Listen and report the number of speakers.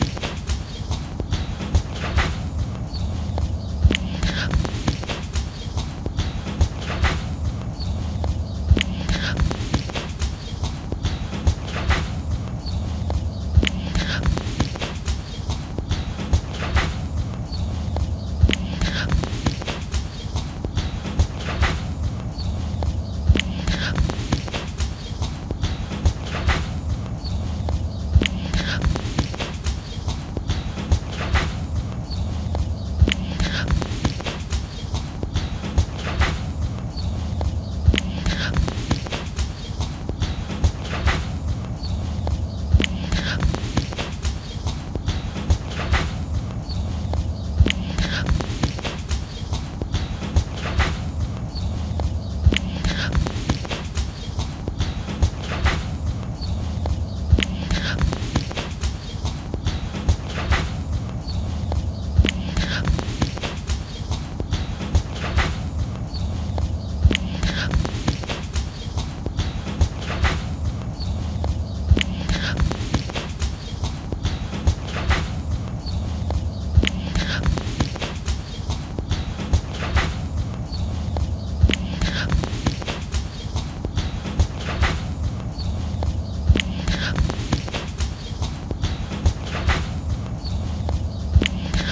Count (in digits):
0